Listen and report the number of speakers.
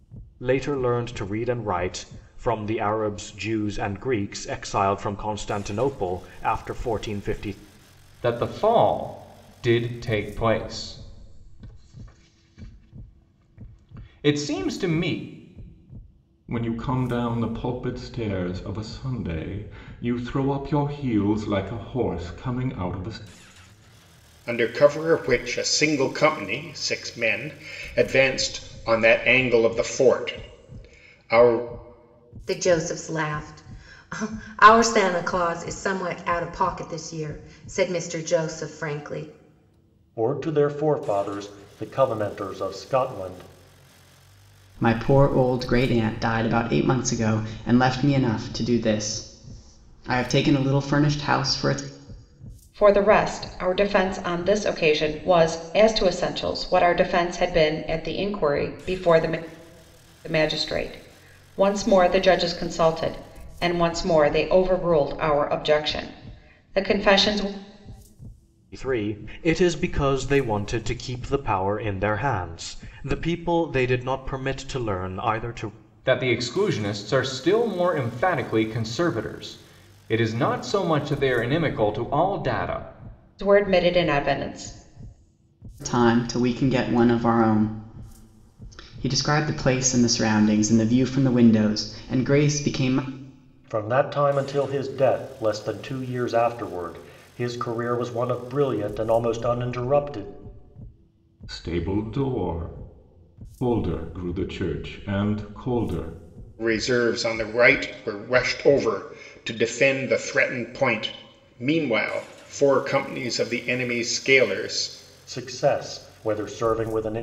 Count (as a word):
eight